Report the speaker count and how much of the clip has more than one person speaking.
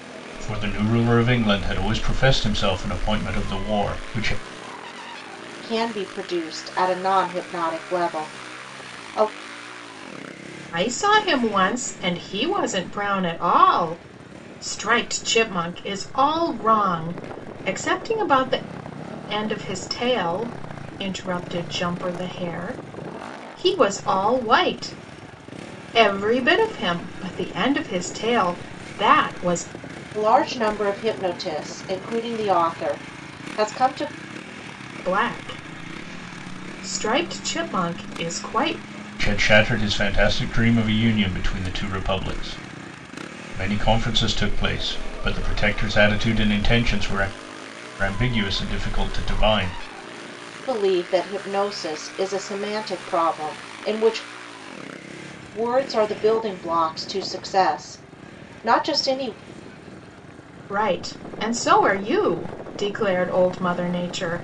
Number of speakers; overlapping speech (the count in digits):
3, no overlap